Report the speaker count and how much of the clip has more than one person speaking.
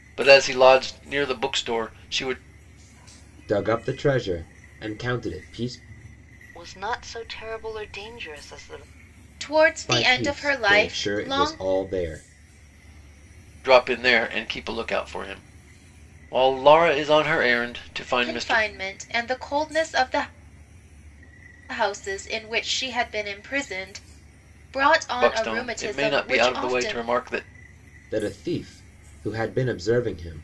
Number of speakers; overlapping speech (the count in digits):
4, about 14%